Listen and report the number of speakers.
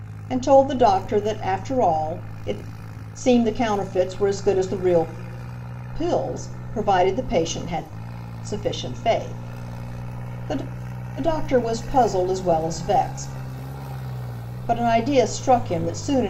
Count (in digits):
1